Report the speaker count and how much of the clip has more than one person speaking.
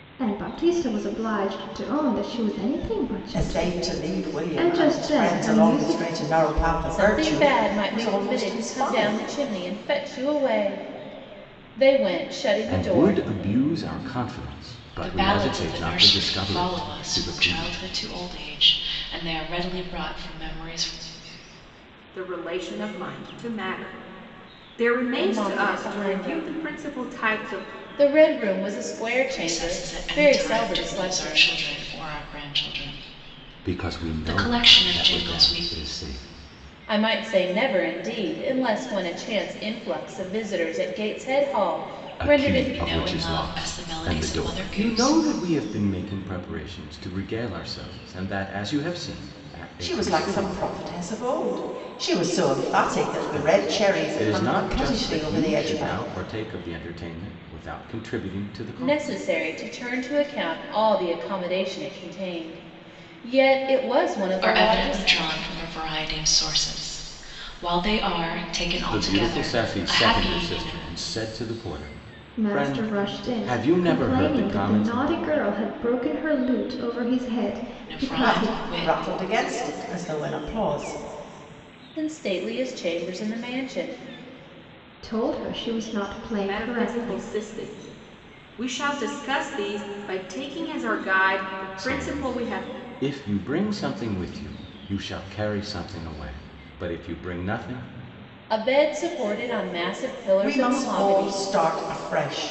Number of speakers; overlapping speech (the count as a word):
six, about 31%